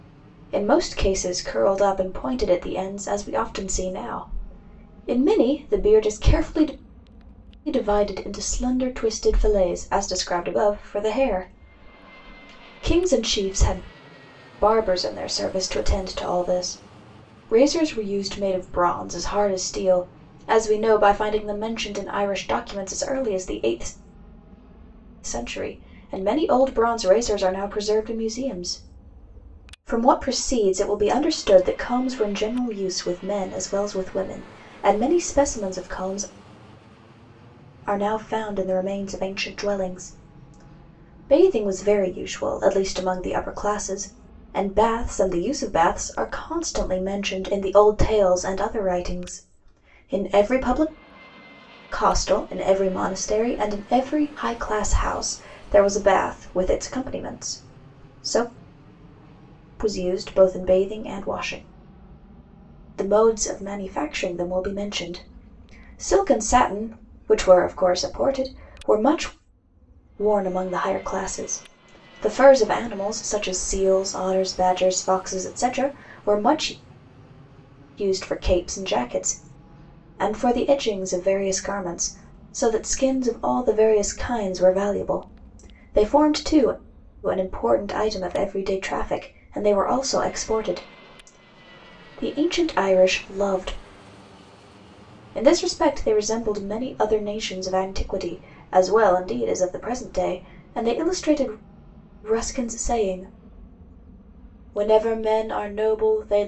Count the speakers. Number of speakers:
1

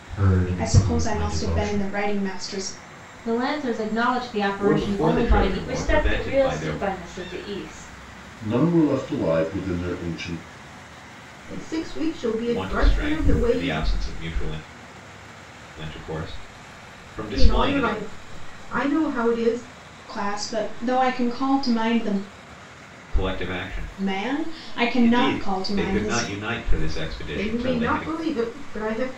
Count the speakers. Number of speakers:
7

